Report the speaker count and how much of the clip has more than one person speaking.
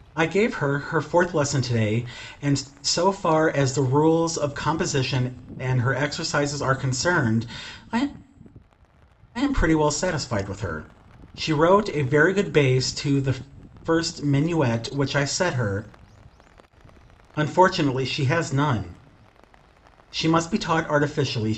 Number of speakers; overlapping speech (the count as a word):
one, no overlap